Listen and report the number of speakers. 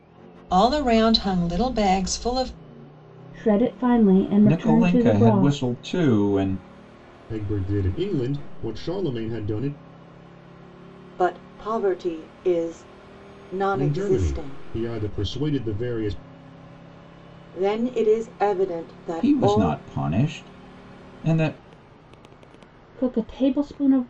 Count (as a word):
five